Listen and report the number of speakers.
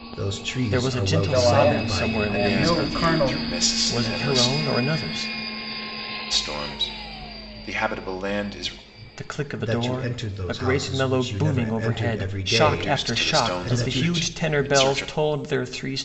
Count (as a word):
four